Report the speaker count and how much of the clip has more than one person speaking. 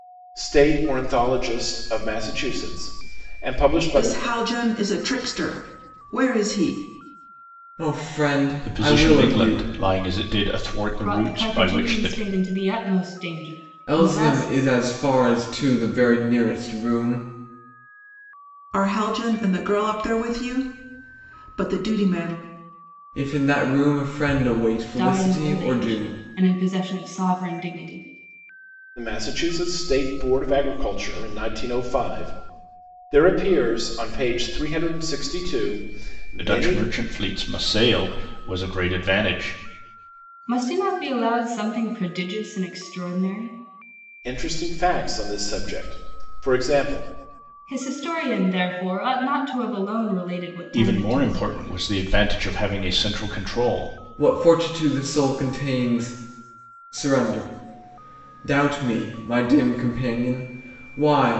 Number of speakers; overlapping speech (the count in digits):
5, about 10%